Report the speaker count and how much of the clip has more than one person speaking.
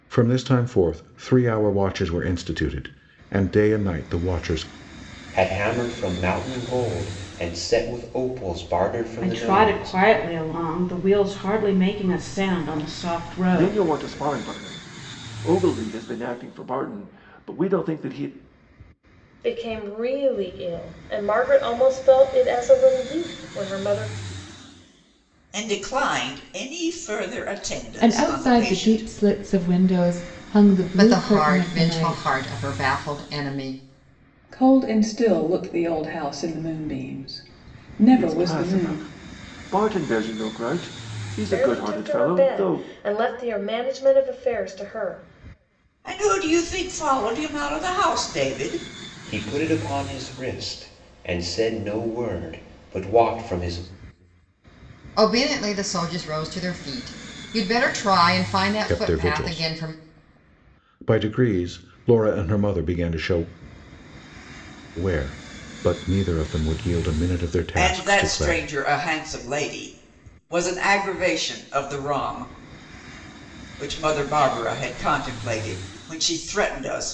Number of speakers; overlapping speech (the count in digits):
9, about 10%